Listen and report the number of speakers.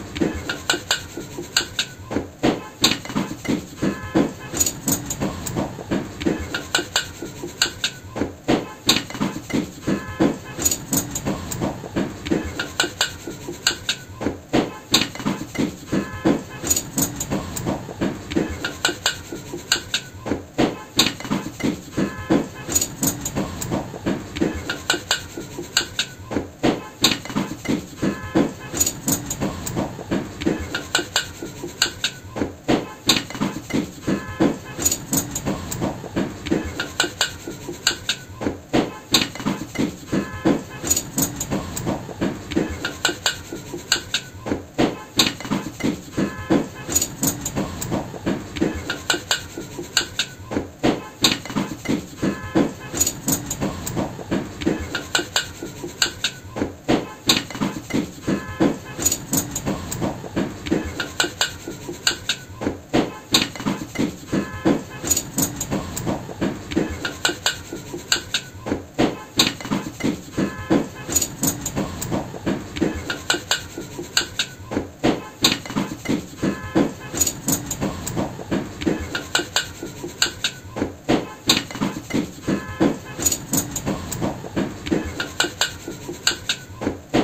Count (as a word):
zero